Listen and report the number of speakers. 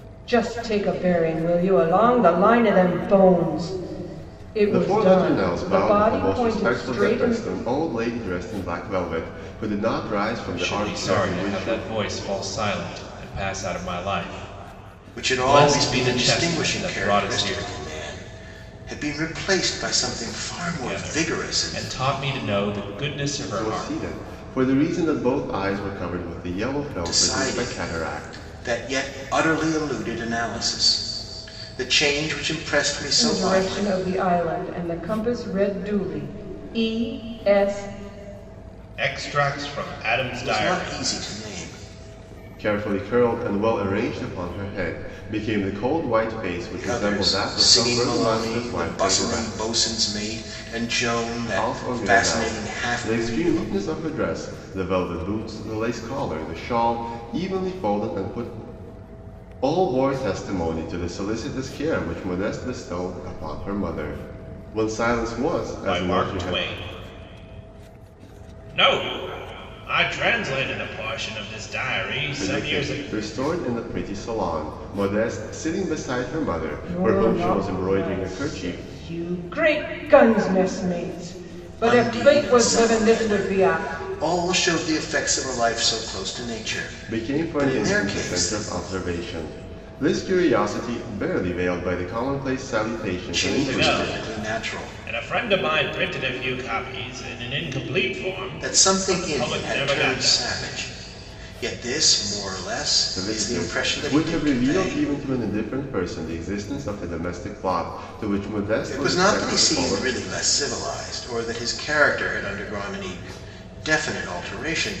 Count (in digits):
4